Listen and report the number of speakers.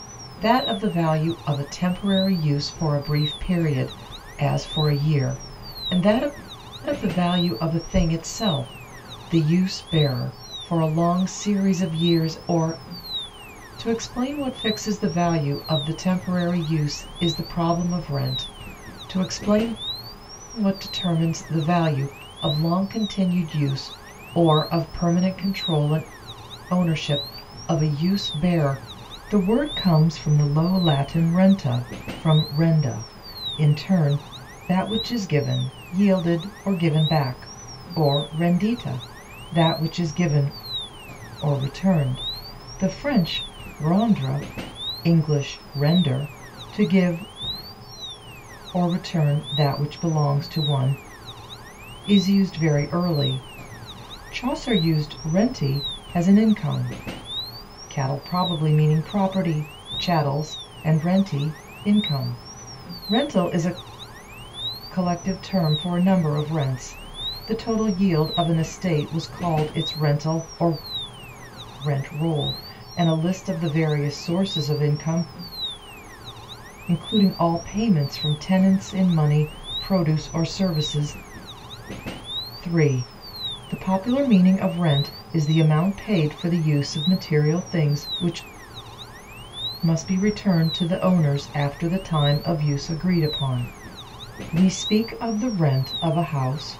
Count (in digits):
1